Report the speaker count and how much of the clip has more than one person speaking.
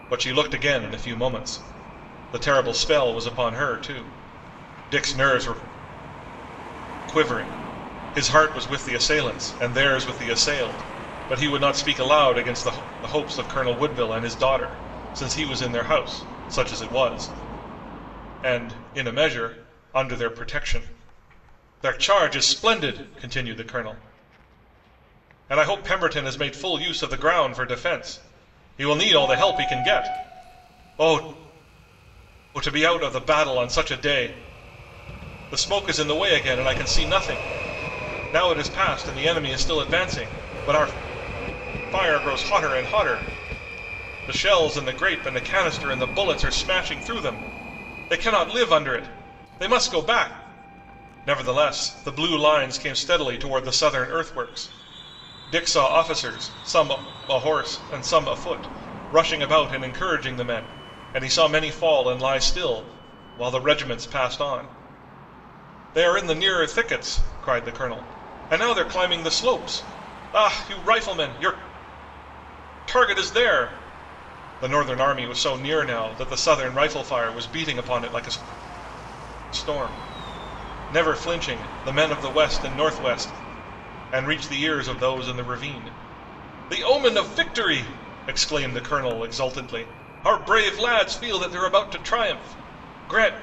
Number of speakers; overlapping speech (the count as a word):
one, no overlap